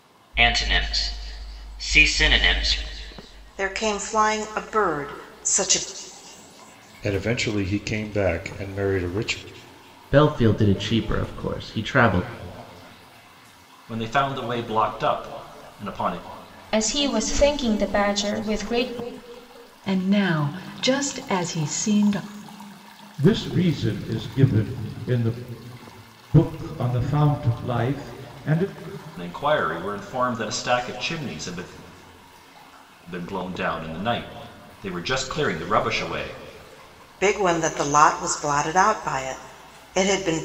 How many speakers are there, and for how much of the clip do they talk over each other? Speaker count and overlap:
eight, no overlap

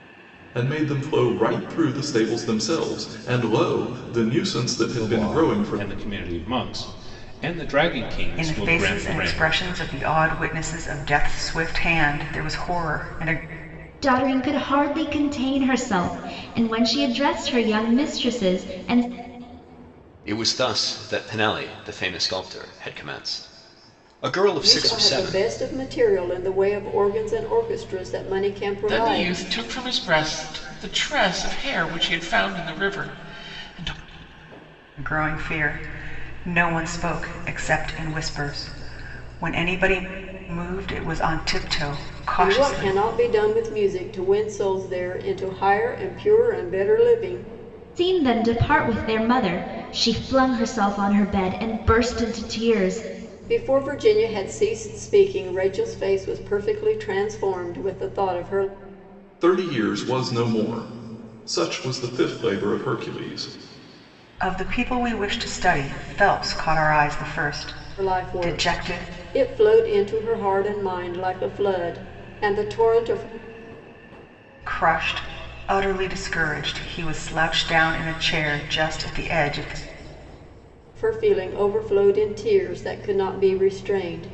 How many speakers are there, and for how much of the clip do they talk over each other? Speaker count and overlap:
seven, about 6%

